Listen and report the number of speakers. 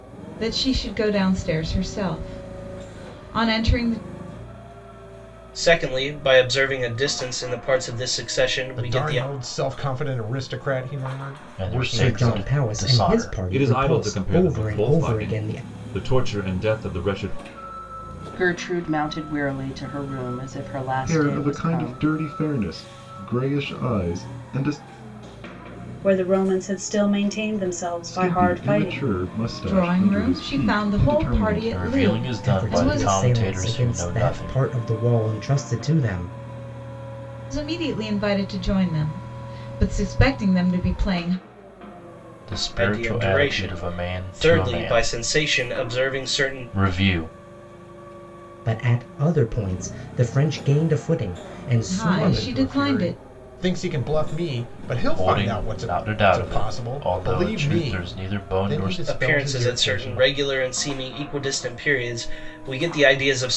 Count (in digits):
9